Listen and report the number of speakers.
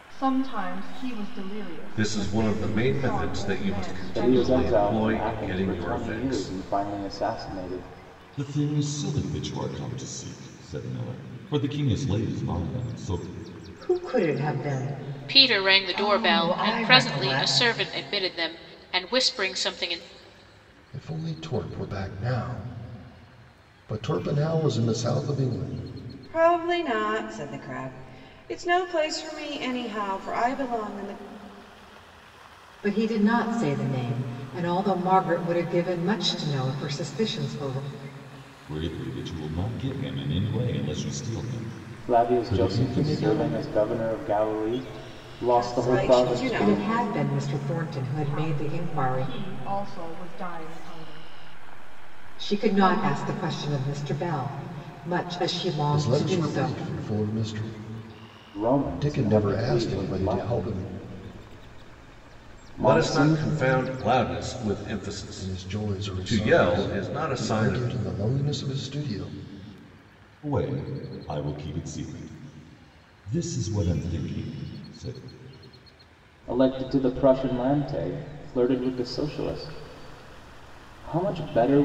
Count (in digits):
8